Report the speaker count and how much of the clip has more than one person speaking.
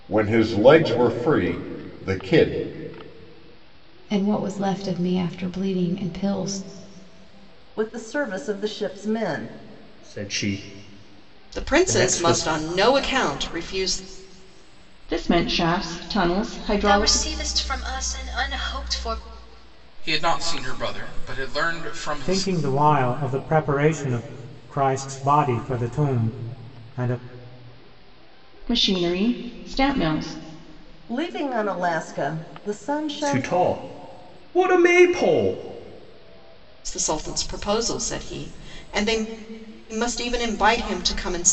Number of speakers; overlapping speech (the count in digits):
9, about 5%